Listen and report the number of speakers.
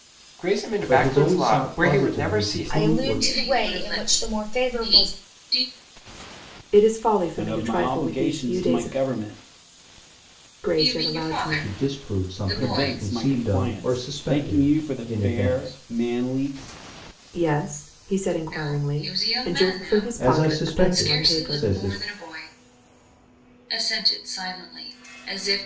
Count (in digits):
6